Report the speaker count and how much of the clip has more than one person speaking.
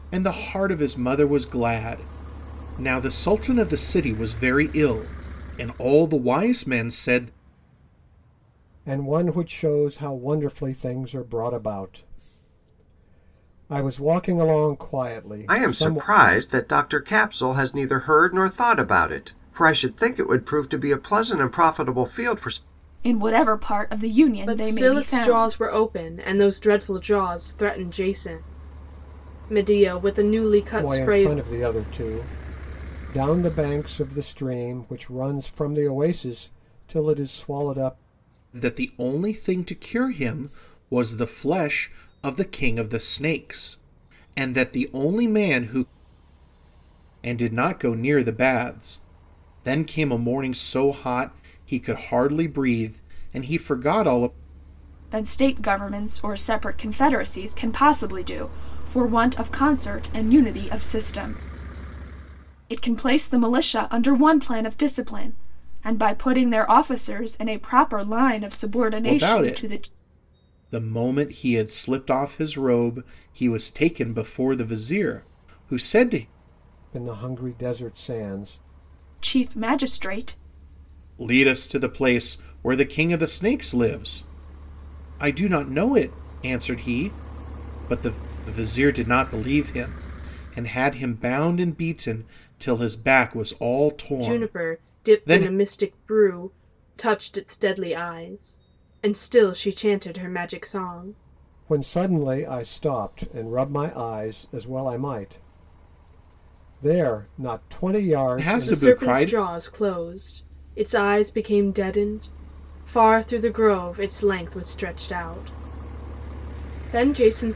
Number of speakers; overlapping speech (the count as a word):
five, about 5%